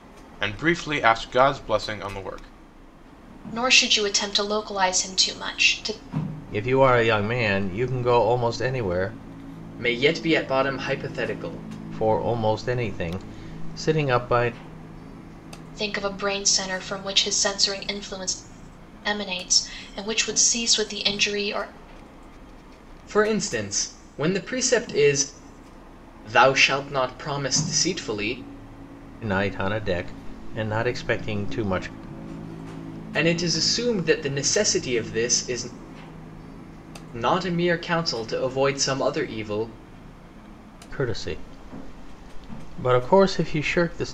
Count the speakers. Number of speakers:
4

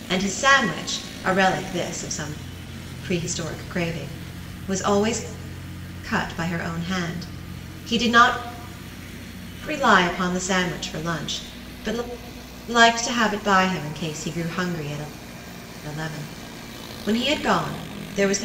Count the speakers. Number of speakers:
1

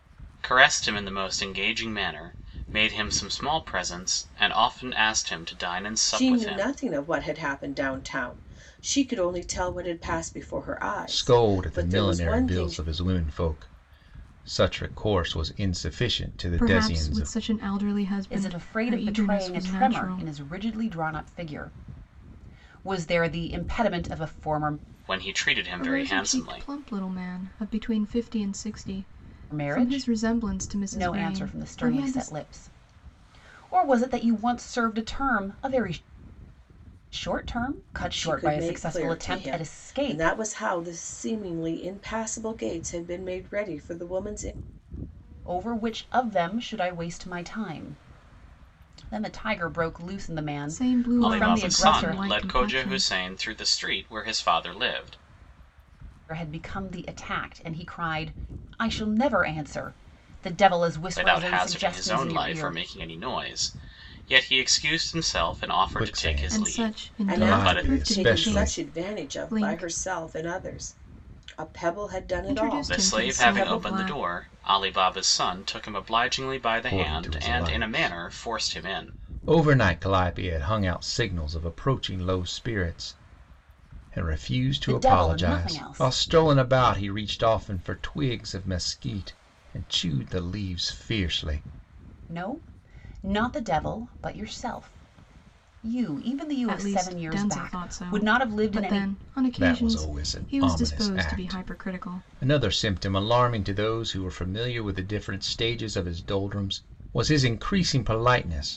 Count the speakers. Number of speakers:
5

